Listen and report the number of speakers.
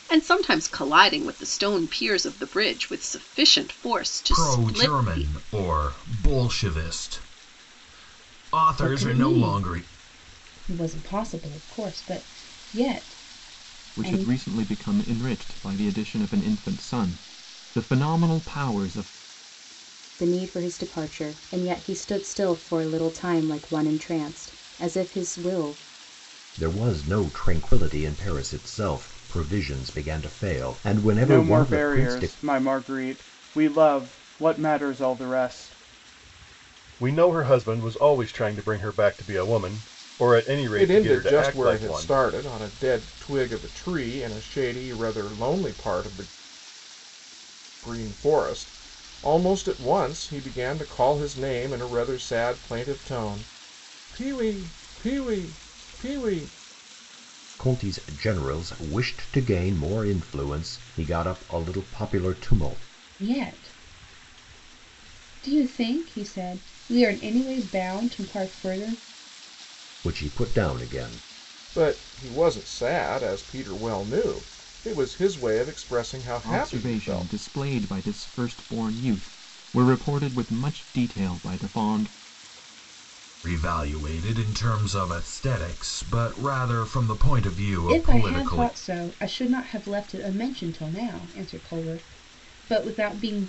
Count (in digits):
9